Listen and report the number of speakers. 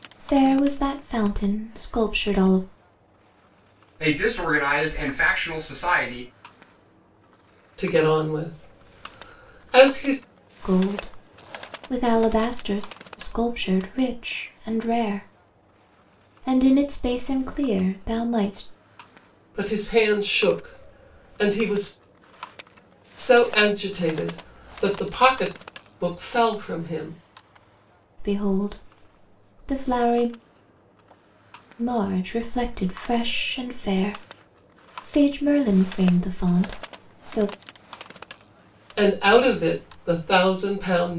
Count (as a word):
three